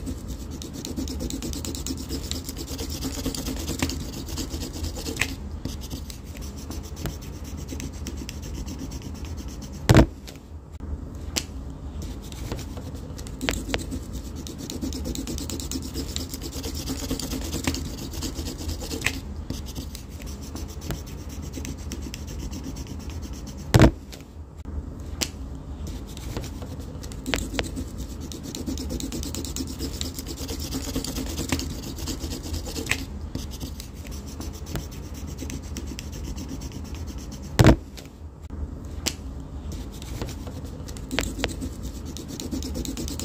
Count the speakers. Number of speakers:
zero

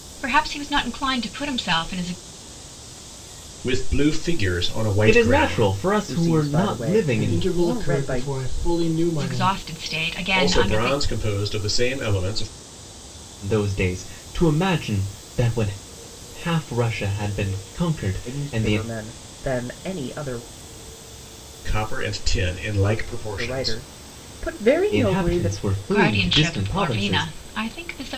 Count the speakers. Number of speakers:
five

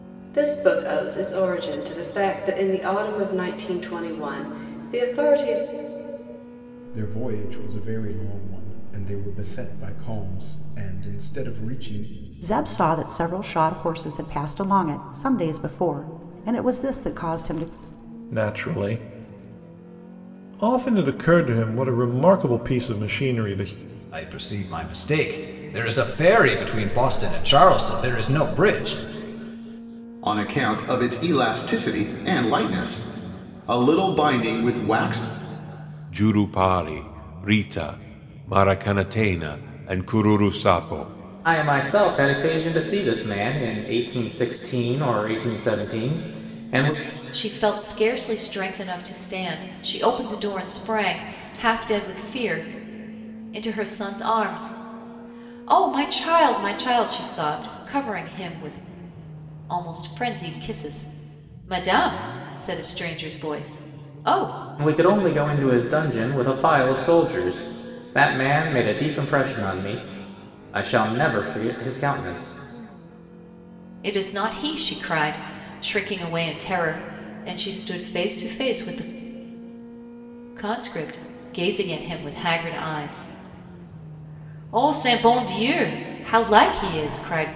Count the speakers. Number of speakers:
nine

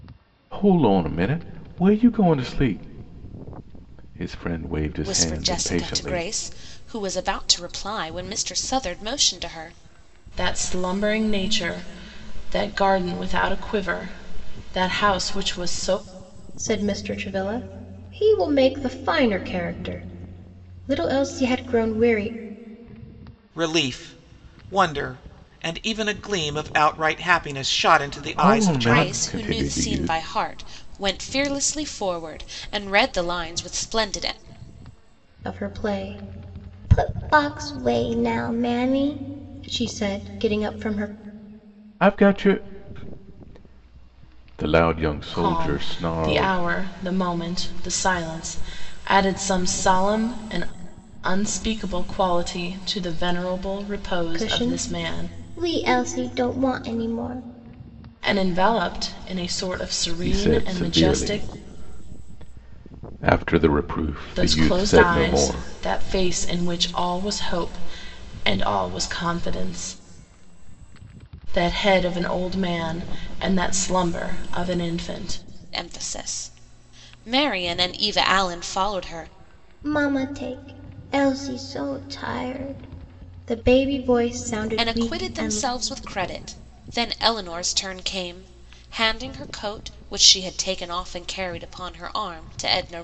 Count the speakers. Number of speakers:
five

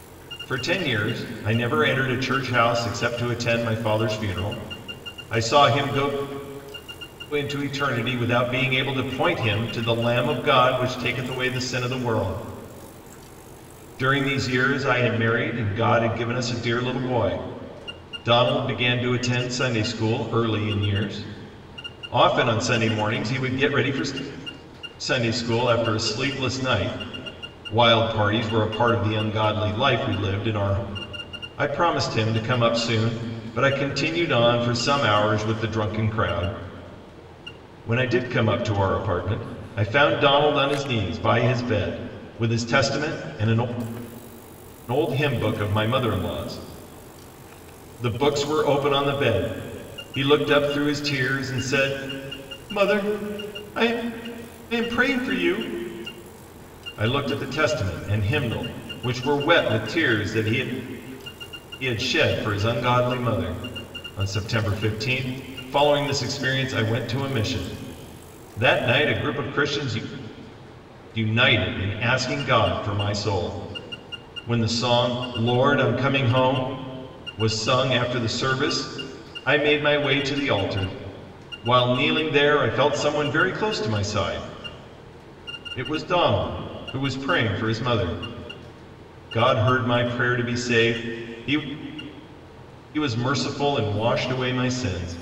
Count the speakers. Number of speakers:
one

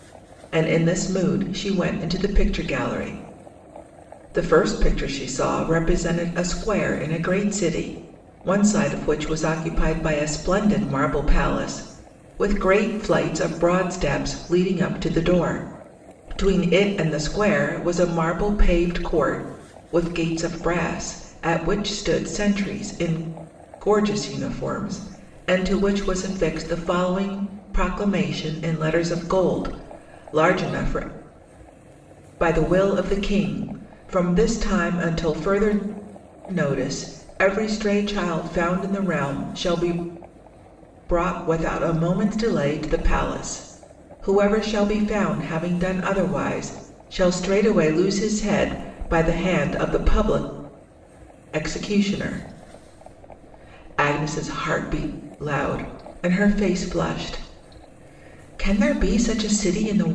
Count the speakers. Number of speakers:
one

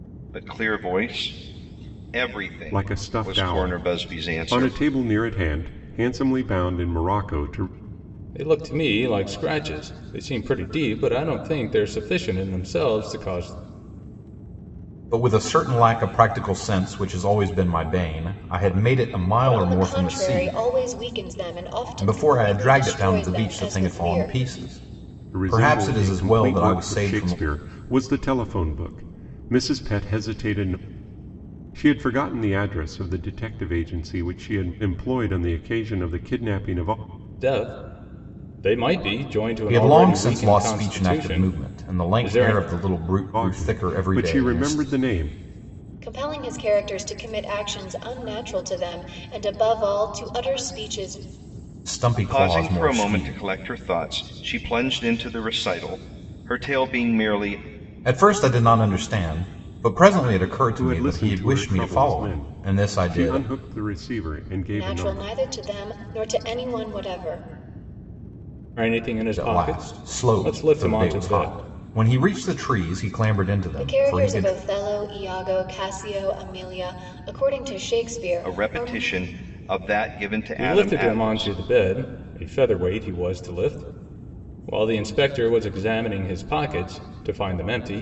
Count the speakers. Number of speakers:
five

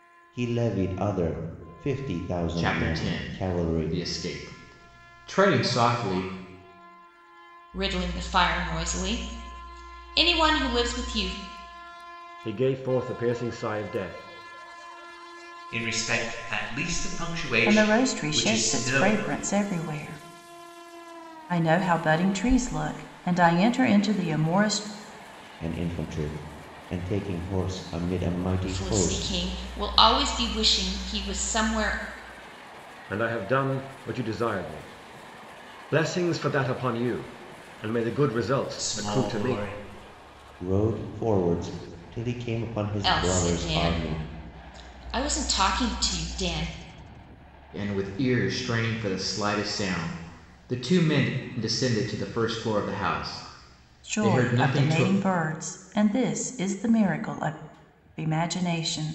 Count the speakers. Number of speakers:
six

